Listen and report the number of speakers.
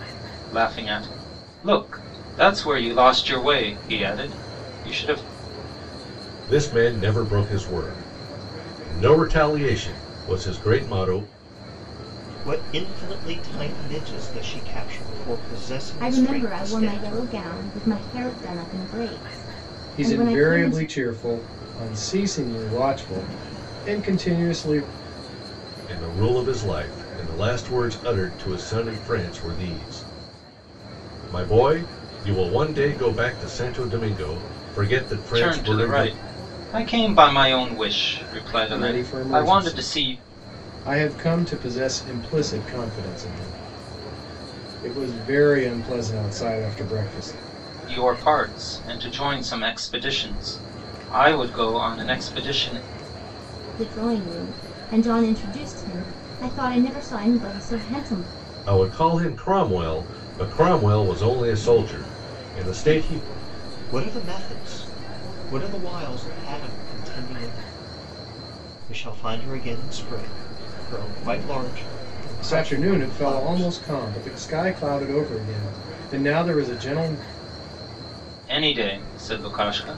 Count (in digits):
5